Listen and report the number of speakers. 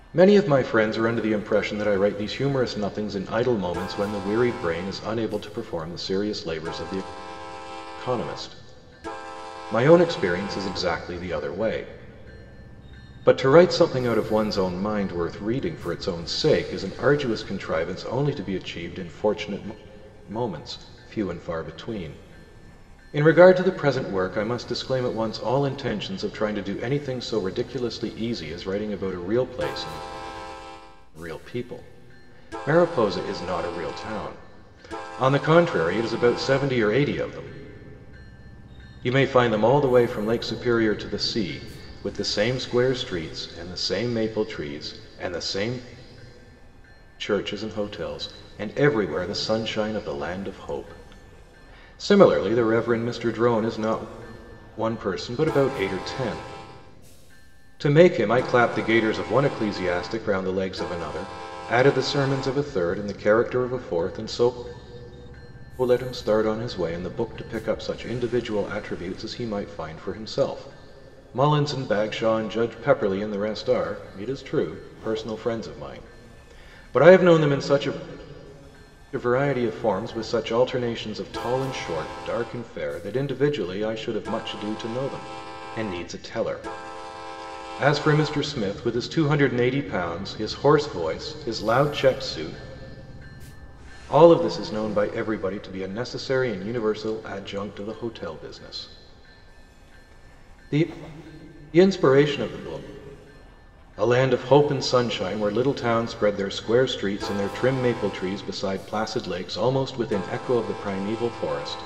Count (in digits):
1